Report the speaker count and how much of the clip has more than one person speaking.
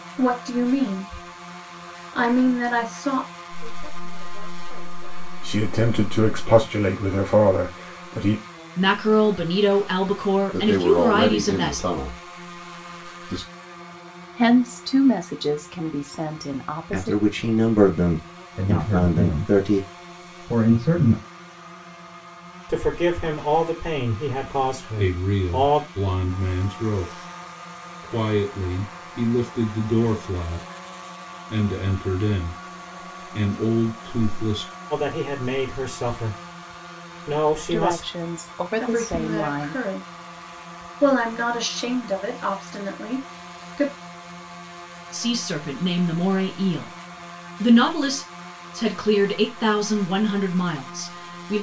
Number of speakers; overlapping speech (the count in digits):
10, about 13%